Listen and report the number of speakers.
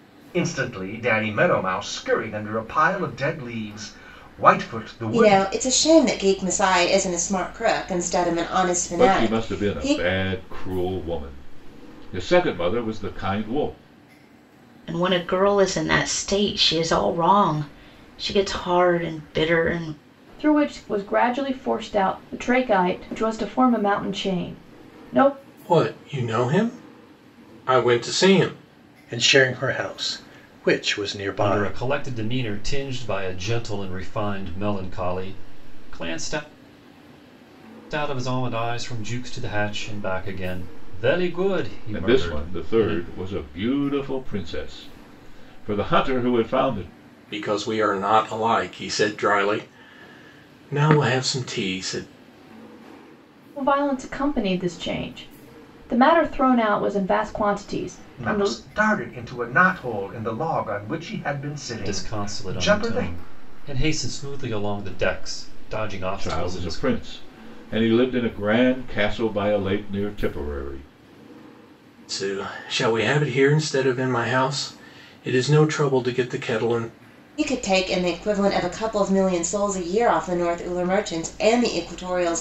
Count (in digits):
8